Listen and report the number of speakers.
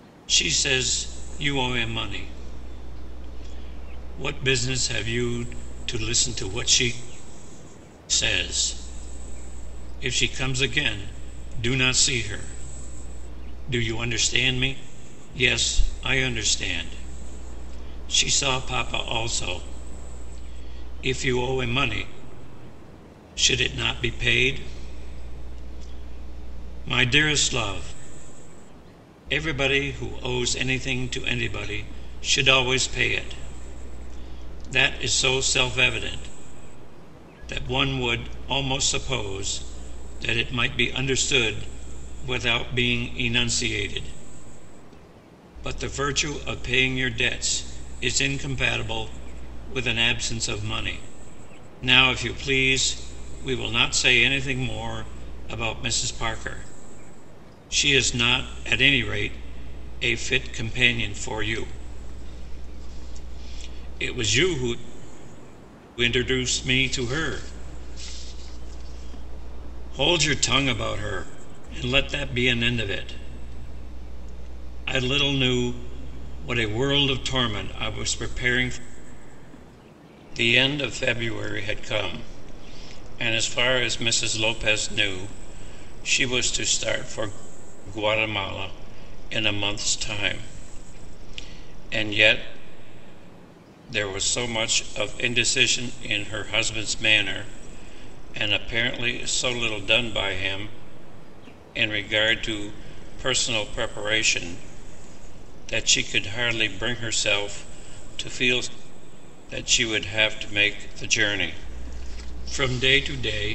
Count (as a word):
one